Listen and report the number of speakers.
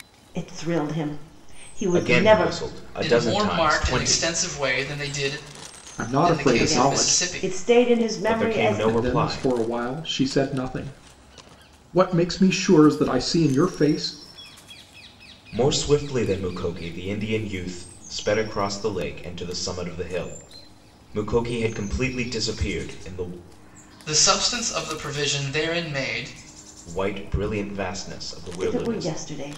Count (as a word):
four